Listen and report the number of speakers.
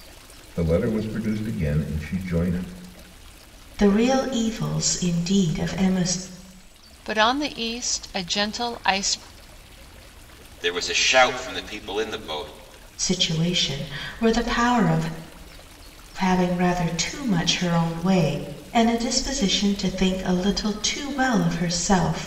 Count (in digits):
4